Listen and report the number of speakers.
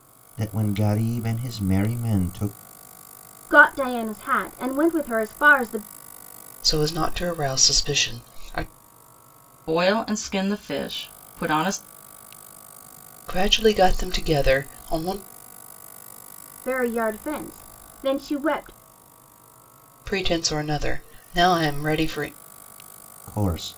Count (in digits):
4